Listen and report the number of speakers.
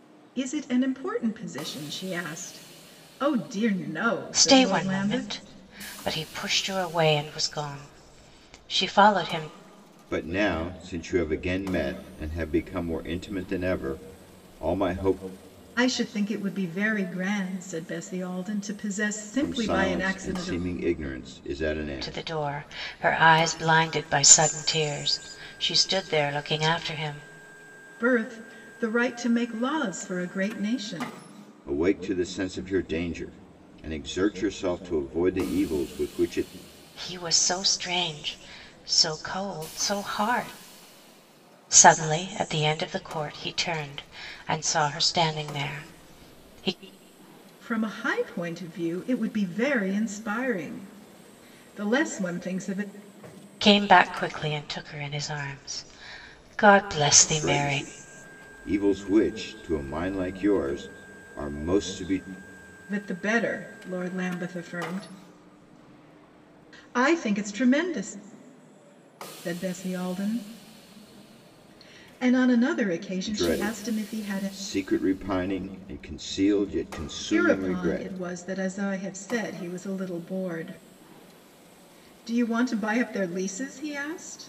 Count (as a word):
three